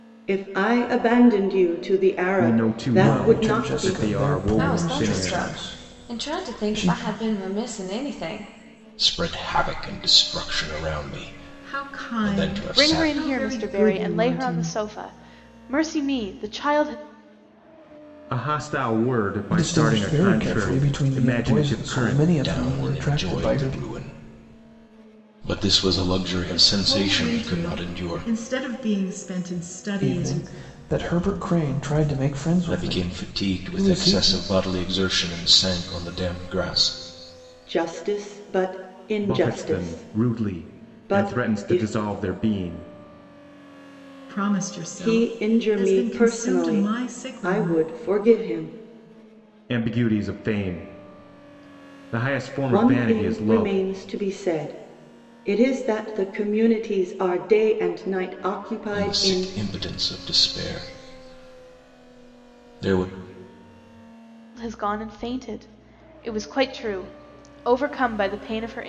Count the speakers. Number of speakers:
7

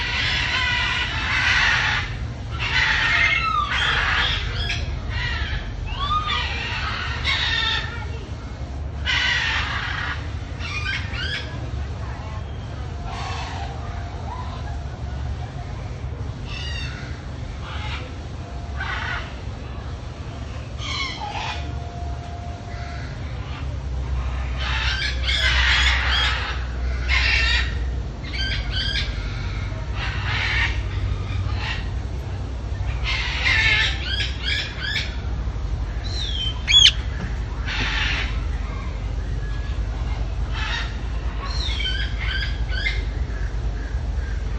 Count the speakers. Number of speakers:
0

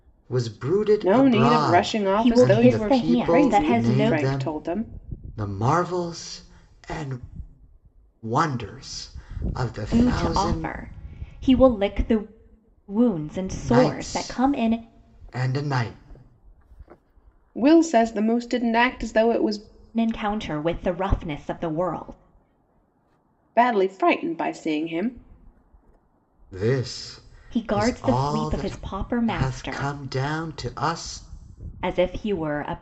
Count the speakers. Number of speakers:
3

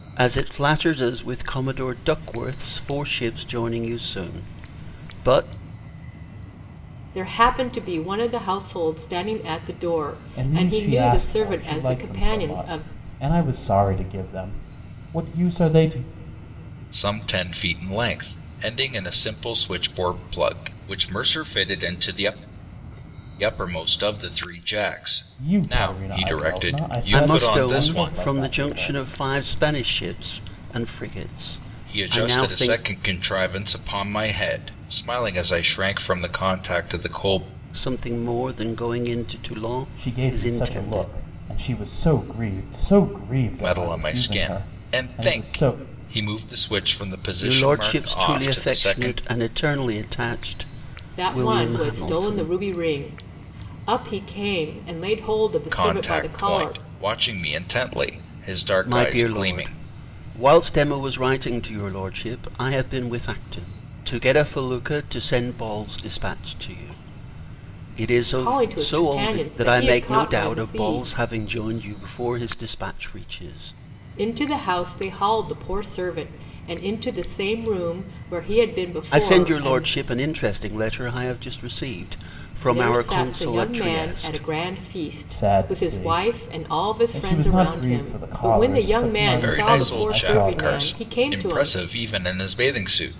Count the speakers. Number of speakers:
4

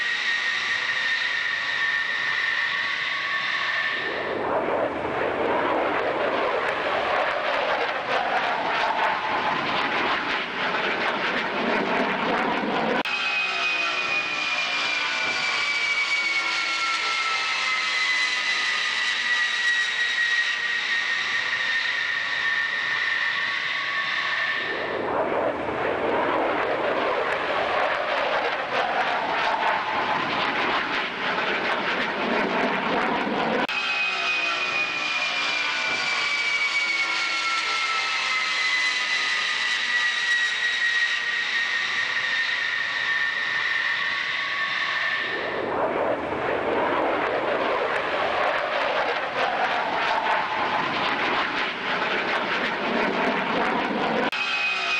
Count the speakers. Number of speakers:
0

